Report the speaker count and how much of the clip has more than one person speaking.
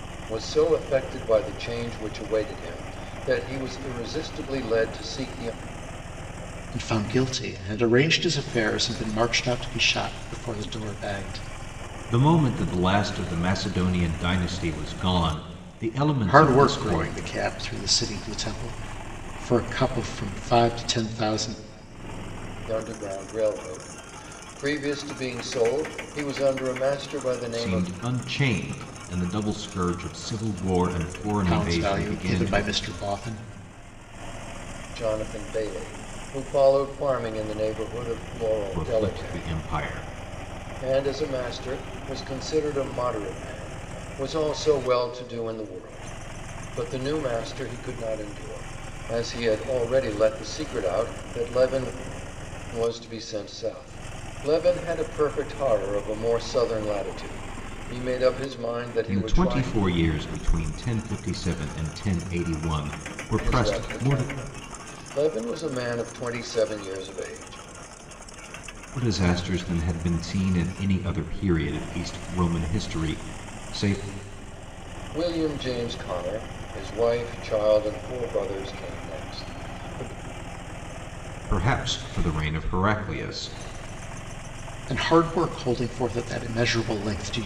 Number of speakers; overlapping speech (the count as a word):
three, about 6%